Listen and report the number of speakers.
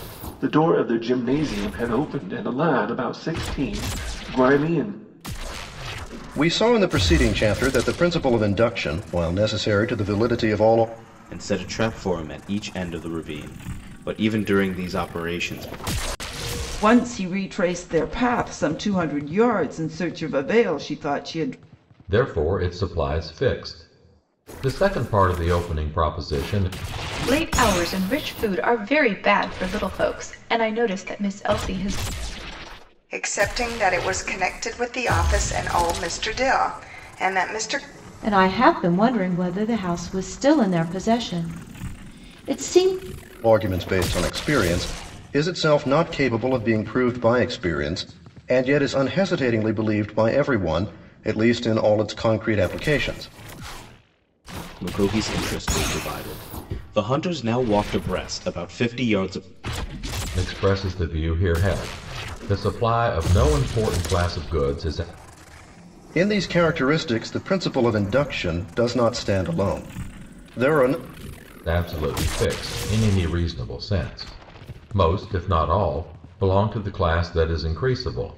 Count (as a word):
eight